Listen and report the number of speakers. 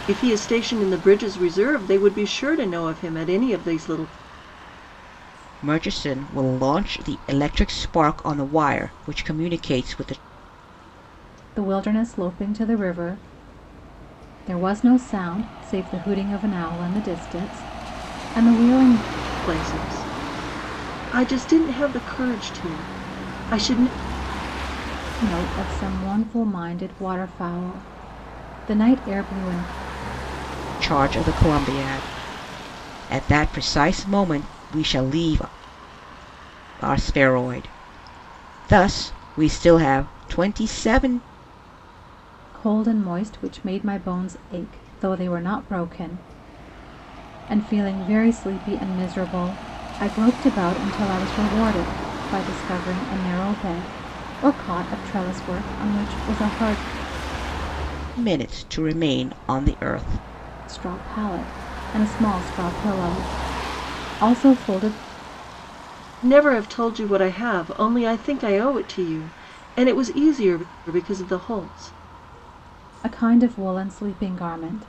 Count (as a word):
three